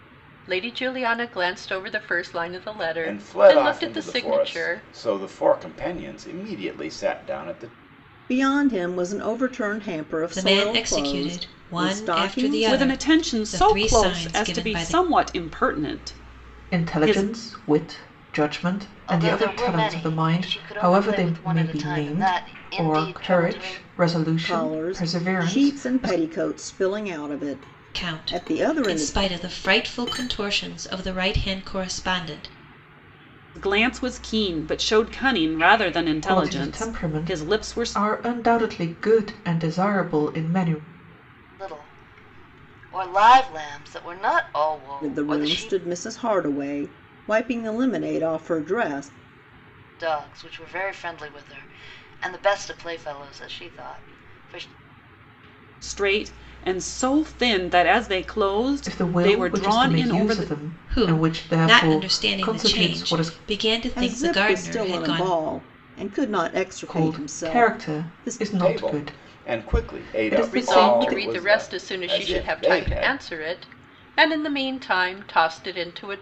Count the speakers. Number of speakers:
7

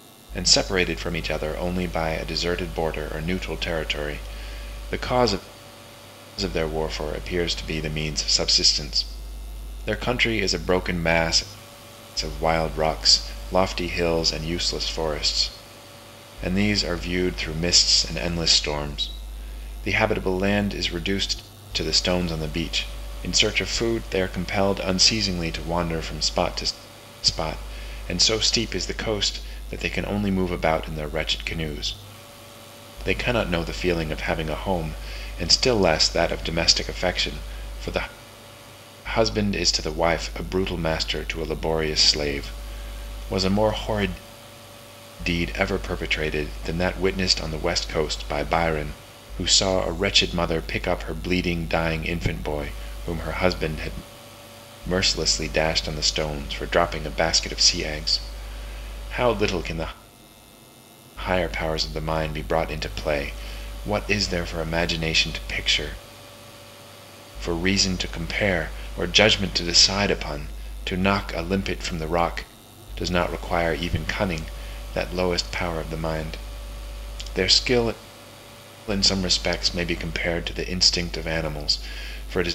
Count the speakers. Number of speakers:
1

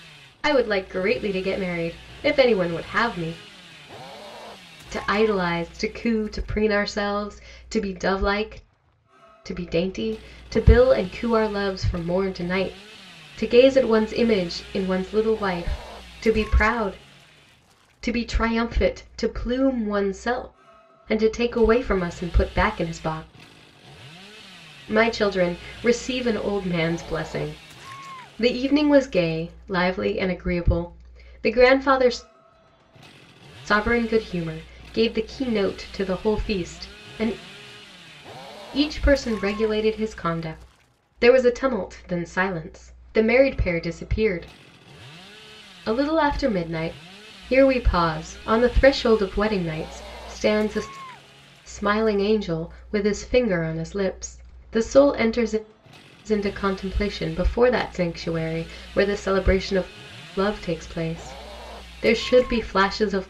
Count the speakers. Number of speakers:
1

